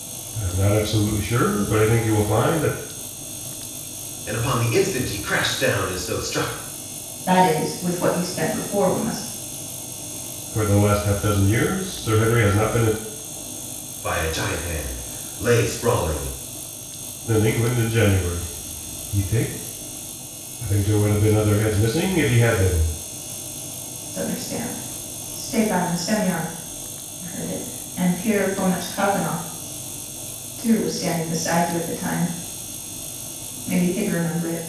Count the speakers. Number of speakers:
3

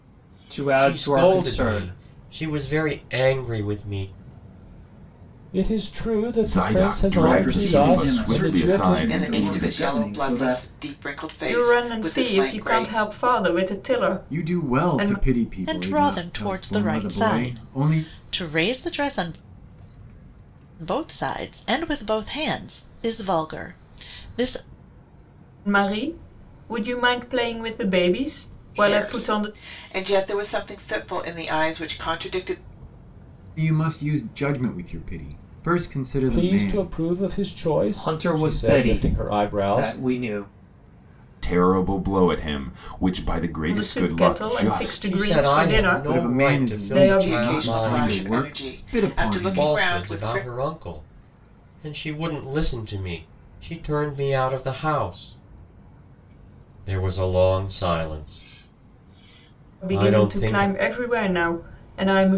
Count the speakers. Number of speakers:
9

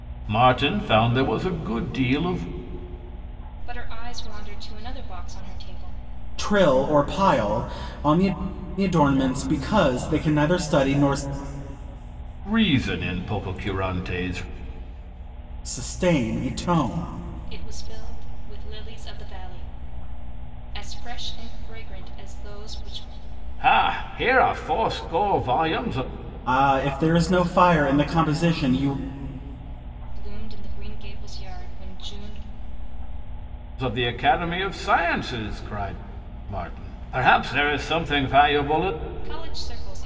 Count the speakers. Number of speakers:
3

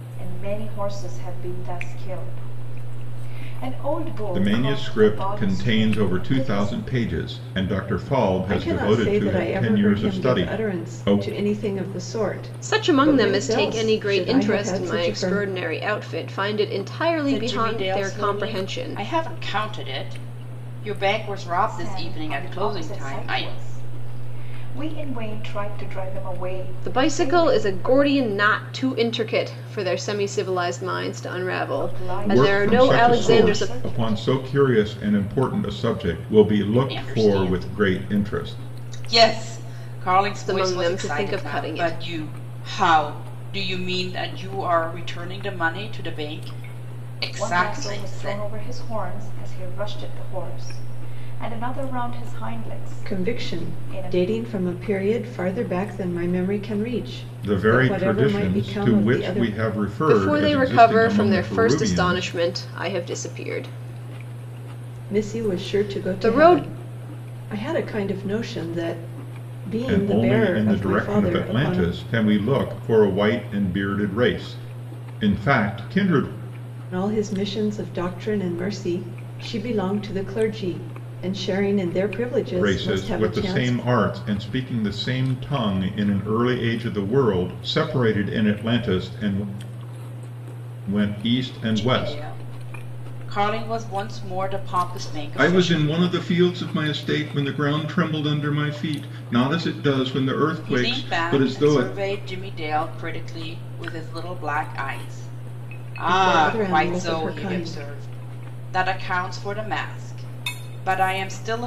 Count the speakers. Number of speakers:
5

